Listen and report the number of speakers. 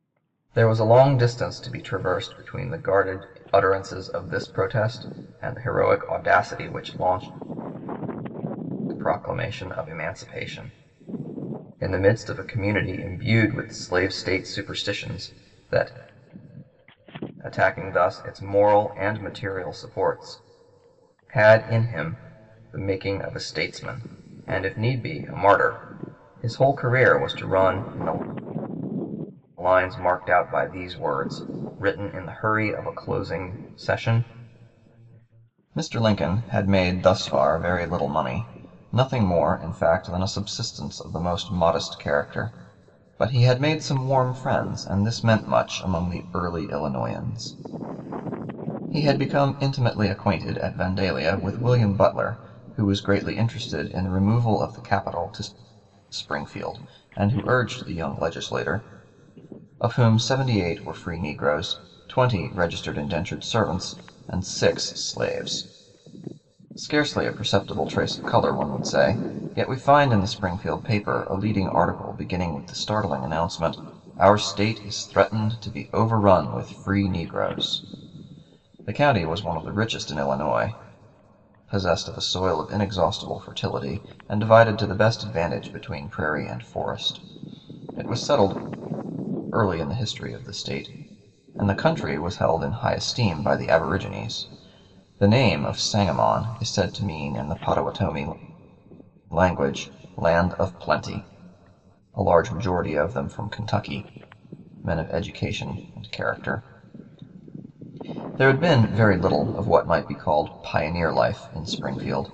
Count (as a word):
one